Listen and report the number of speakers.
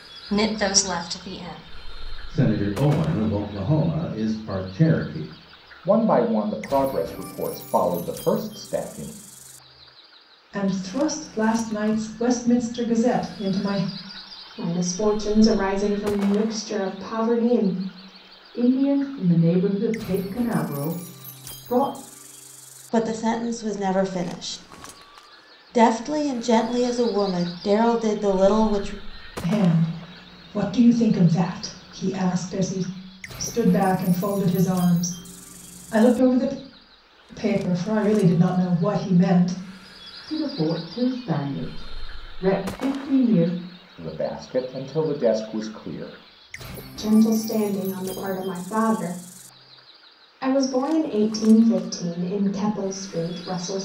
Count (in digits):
7